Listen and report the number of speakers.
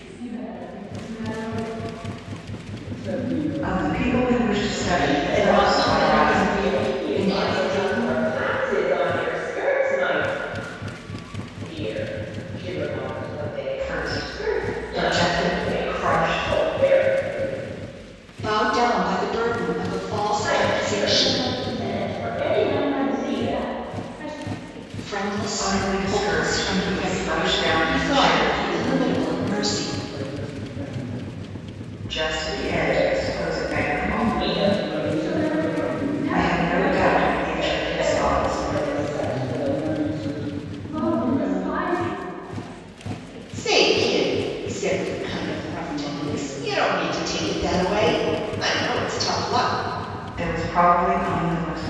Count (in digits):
5